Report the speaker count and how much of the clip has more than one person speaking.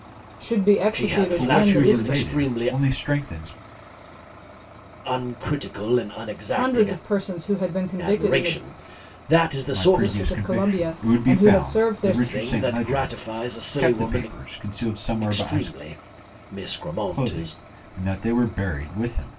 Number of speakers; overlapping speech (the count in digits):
3, about 42%